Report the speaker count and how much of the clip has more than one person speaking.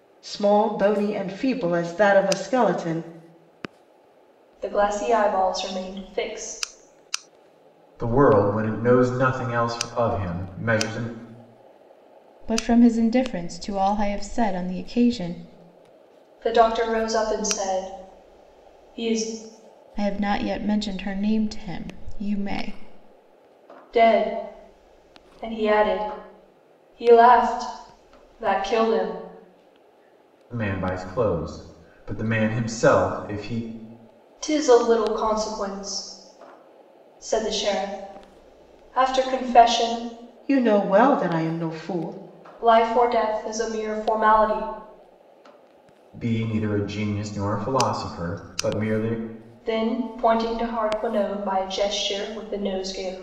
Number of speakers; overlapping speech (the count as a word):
four, no overlap